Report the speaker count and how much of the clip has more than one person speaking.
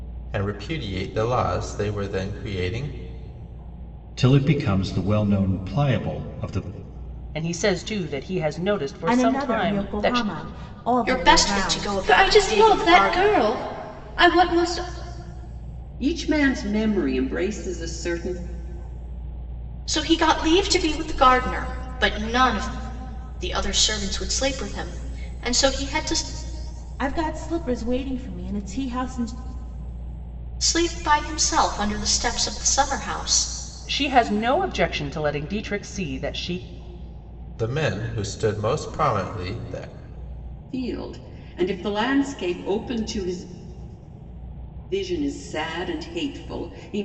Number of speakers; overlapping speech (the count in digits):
7, about 8%